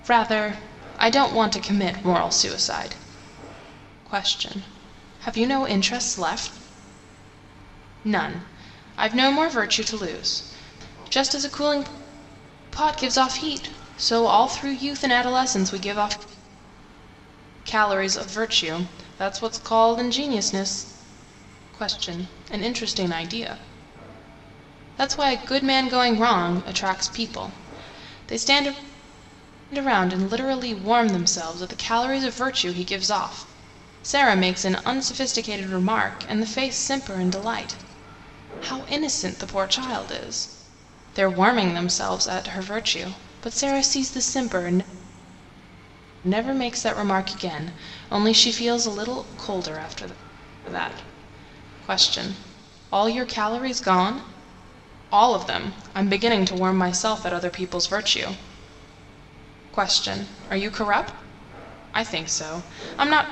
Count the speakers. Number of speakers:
1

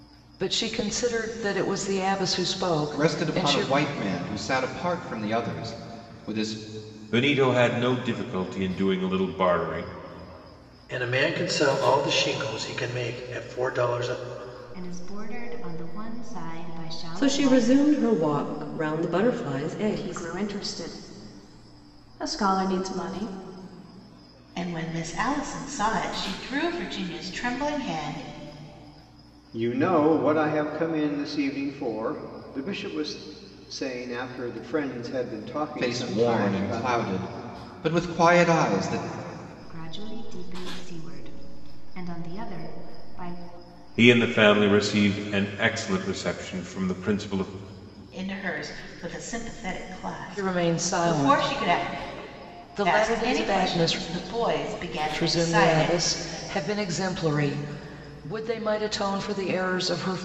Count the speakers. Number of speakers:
9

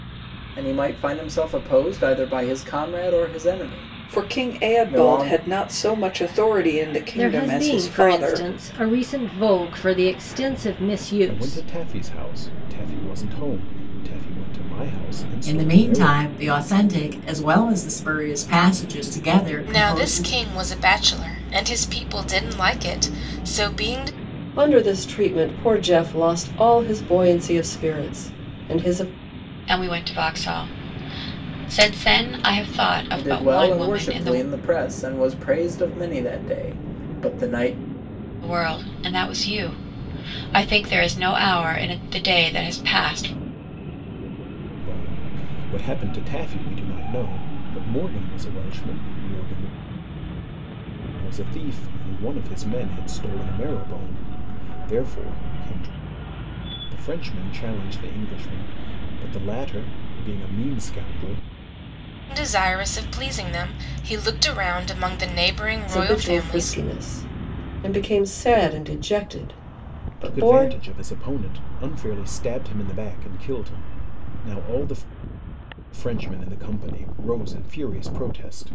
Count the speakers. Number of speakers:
8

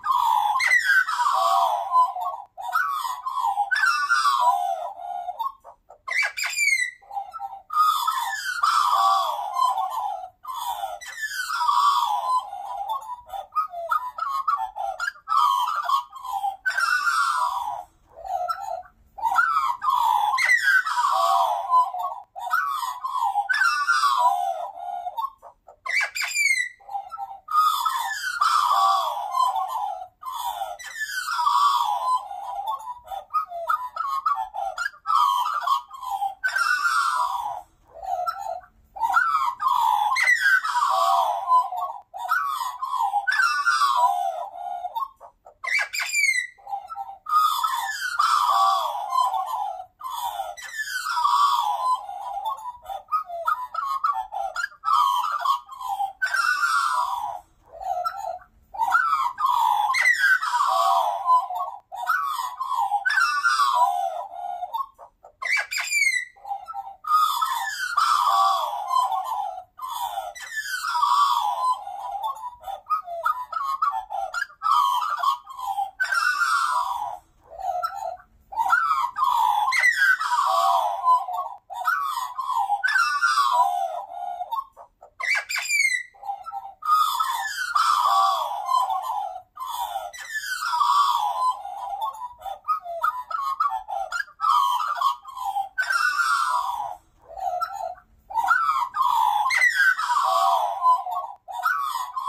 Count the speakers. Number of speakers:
0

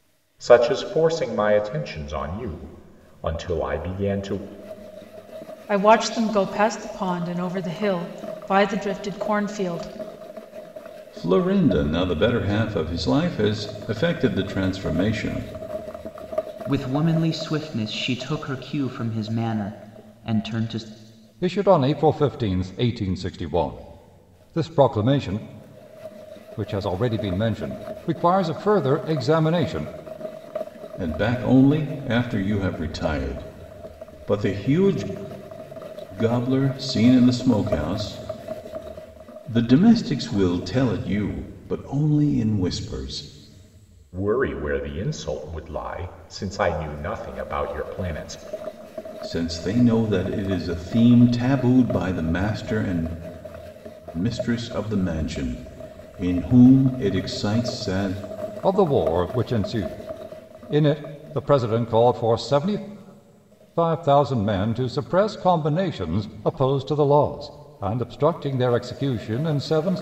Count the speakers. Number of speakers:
5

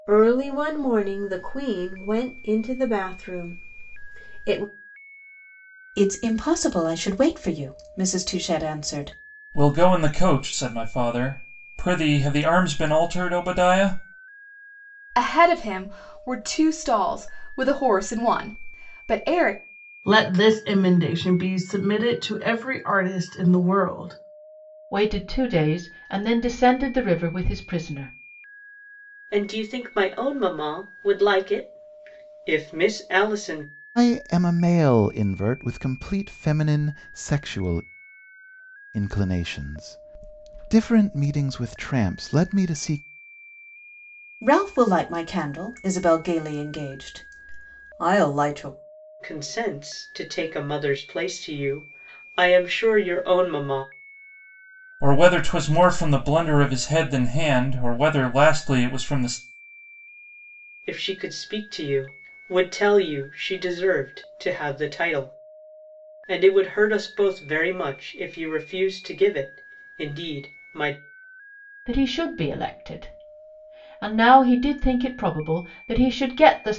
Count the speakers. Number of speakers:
8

